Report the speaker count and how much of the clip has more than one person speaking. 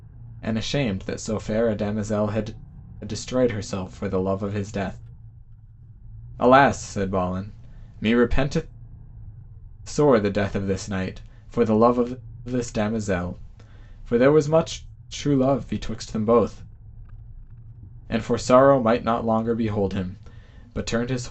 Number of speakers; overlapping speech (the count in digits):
1, no overlap